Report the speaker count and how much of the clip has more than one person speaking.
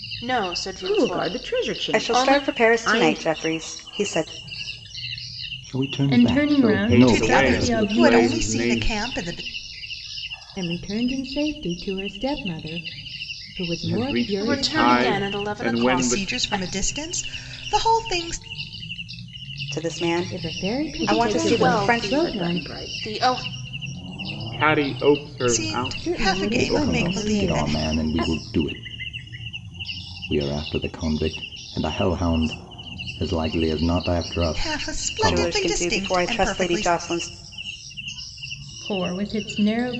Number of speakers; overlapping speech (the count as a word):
eight, about 41%